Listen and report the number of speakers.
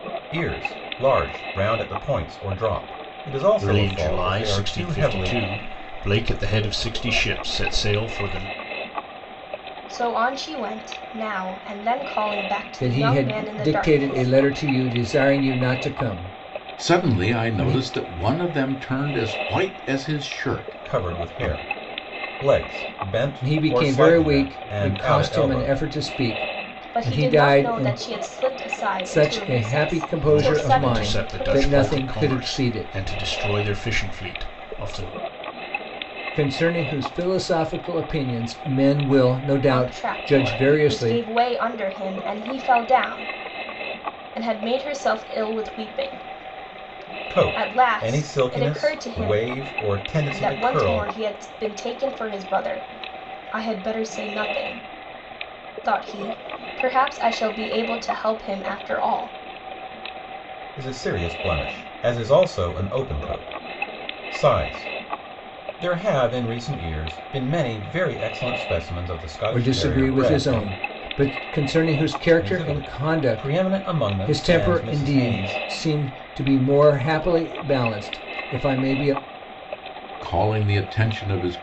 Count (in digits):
5